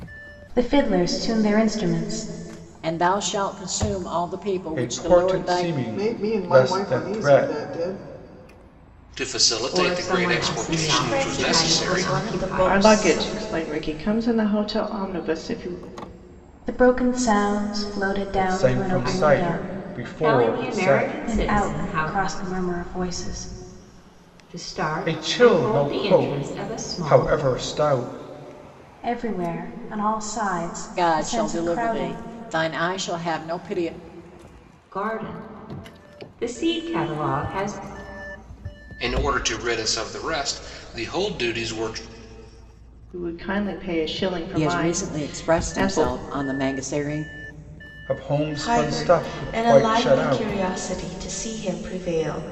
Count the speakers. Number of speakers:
8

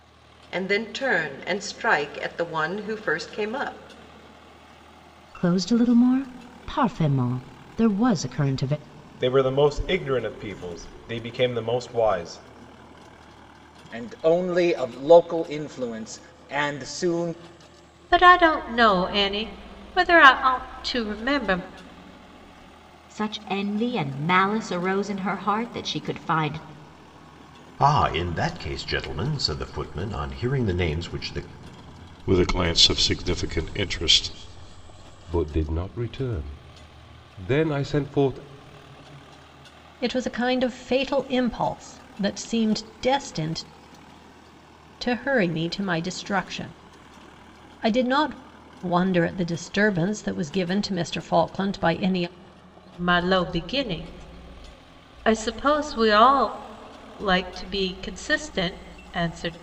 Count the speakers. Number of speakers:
10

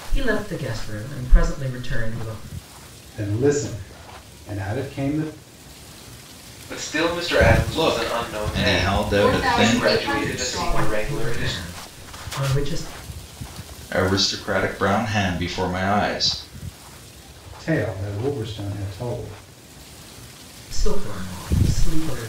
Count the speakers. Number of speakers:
5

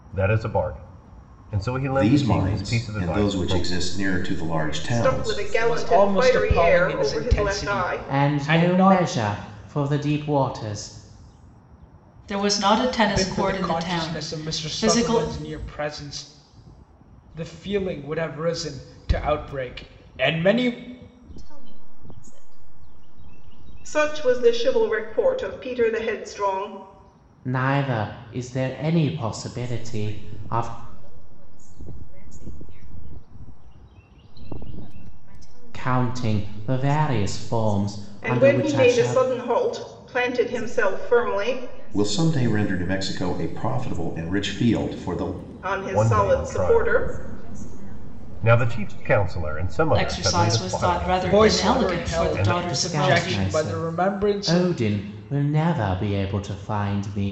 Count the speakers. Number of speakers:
7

